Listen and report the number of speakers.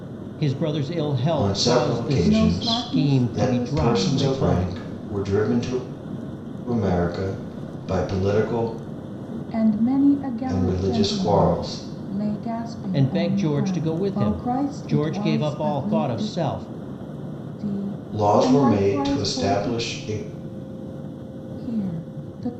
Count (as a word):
three